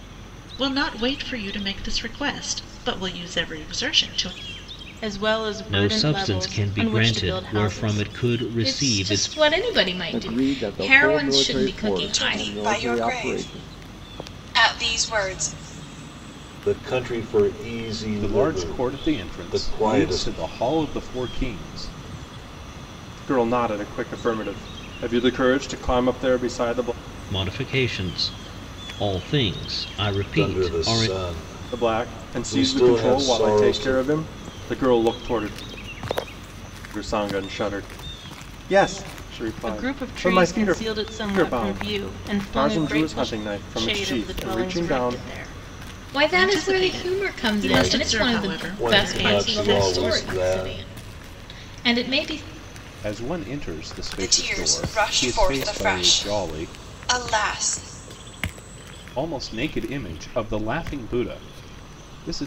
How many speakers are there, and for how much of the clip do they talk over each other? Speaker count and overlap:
9, about 39%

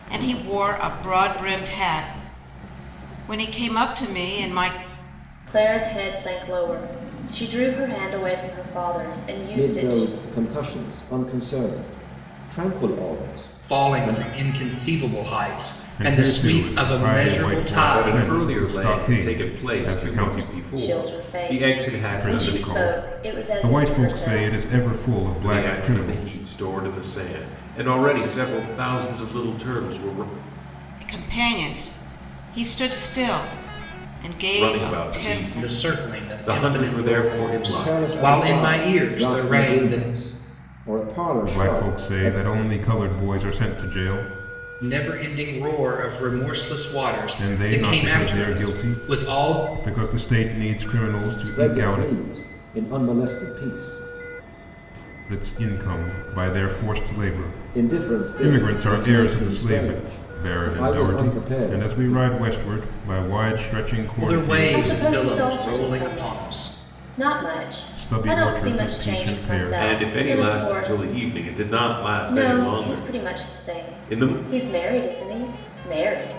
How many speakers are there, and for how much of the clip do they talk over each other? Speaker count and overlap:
6, about 42%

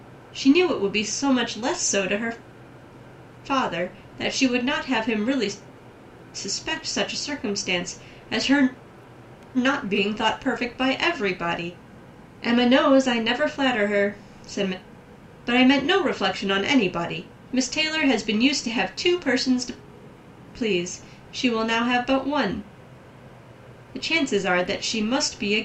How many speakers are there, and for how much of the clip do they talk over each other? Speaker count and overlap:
1, no overlap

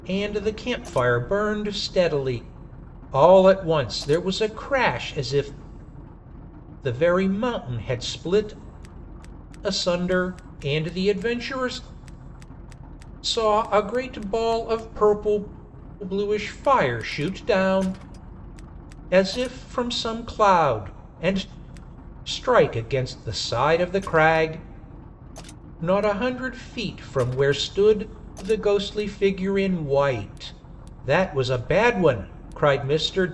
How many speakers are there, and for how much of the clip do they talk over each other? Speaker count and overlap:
1, no overlap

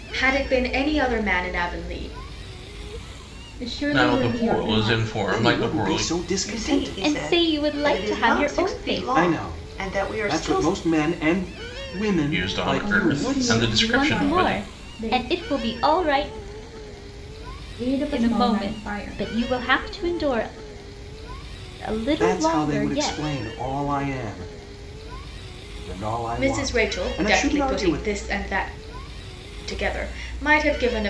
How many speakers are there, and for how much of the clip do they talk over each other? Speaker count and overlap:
6, about 43%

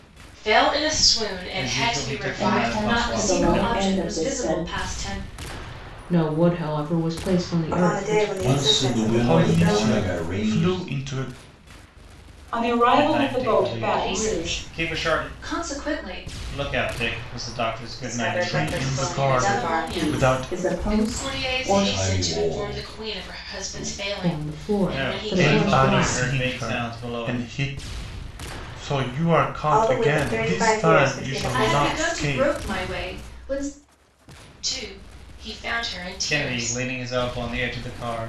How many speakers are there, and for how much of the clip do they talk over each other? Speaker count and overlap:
9, about 56%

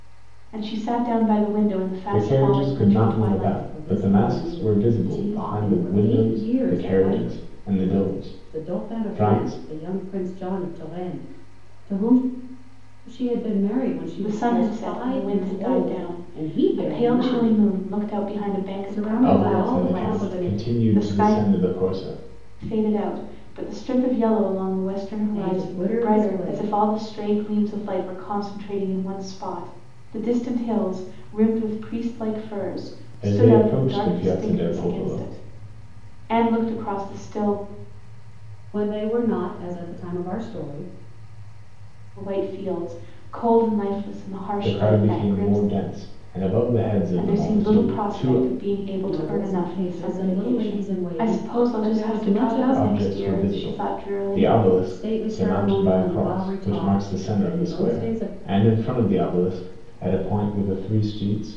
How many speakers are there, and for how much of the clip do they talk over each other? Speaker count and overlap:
3, about 46%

